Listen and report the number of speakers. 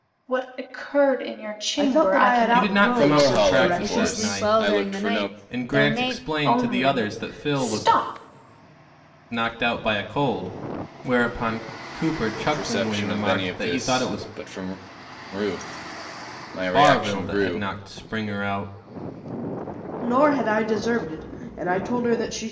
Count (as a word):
five